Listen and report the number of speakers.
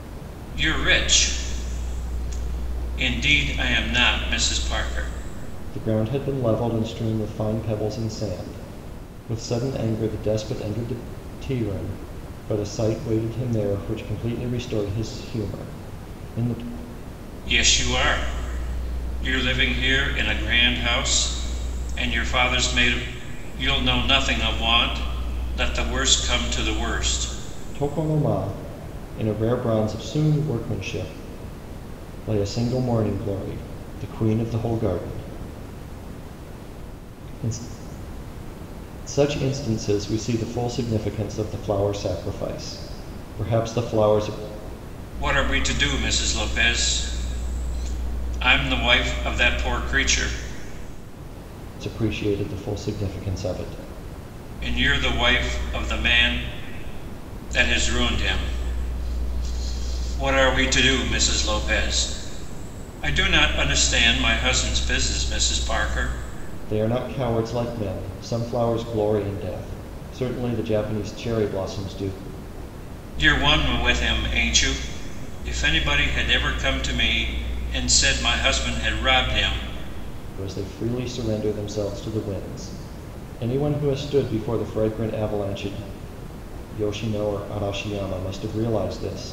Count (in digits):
2